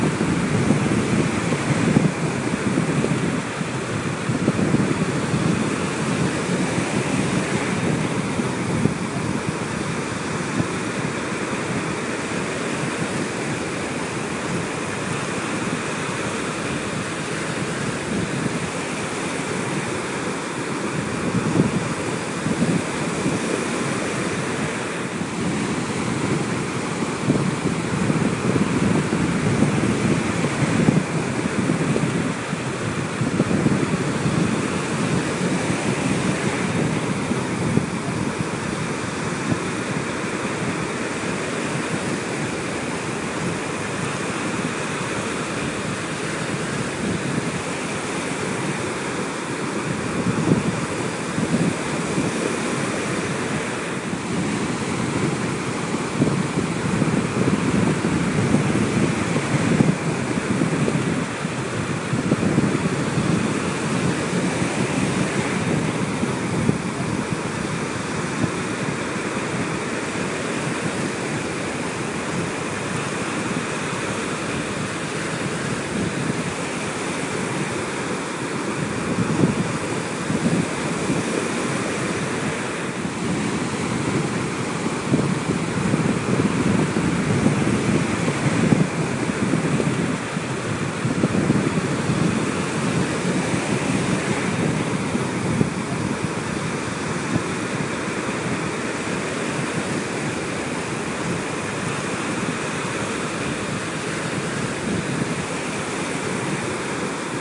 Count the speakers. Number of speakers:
zero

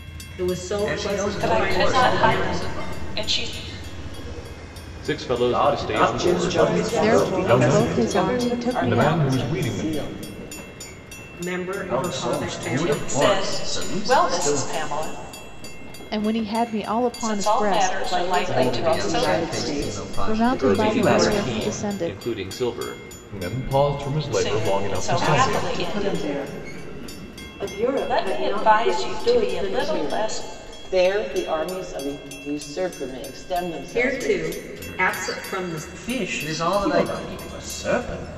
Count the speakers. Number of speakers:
ten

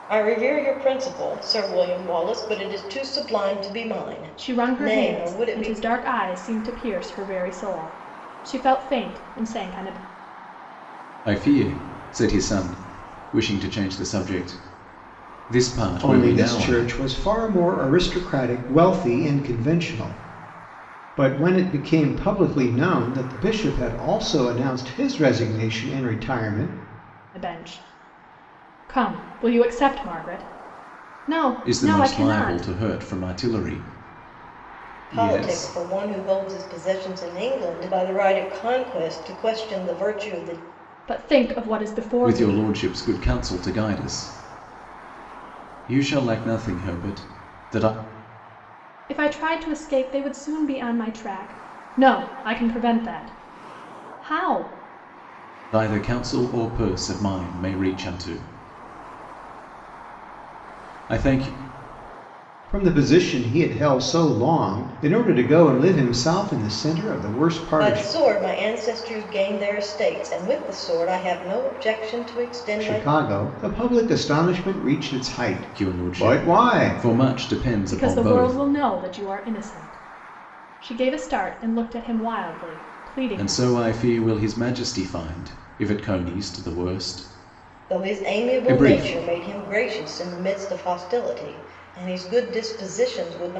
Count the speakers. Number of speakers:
four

